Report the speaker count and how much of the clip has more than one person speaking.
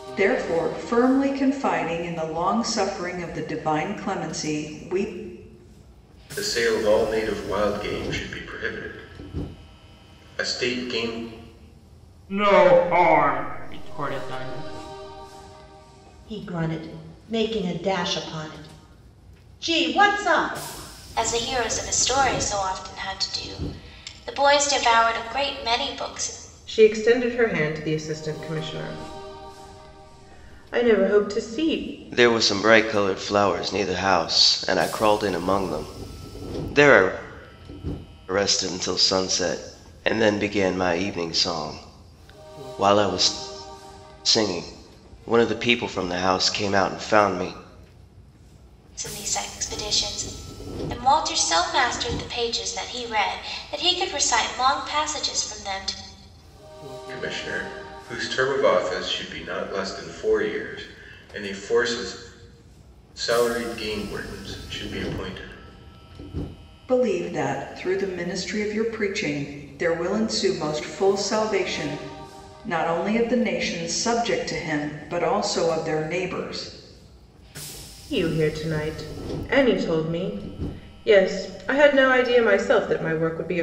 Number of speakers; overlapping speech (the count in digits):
7, no overlap